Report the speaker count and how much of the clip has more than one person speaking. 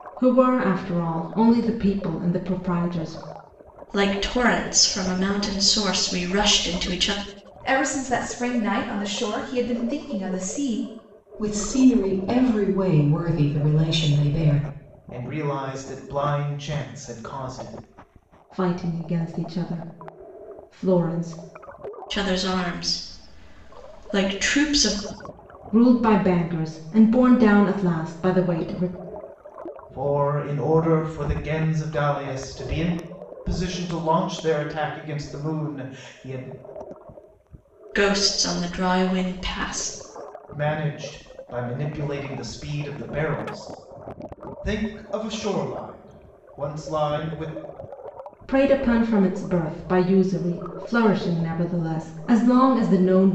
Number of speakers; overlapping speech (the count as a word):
five, no overlap